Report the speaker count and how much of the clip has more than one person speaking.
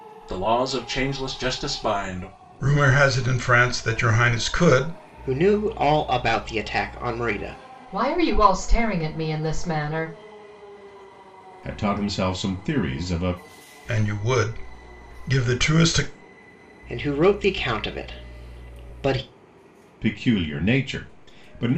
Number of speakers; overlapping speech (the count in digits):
5, no overlap